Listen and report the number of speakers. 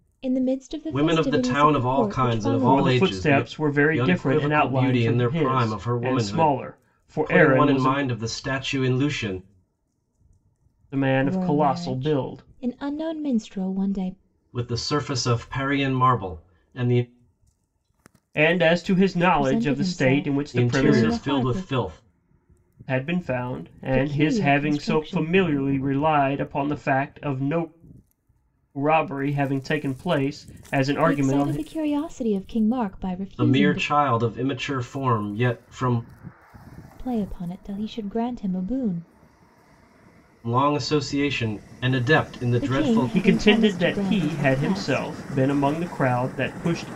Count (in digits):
3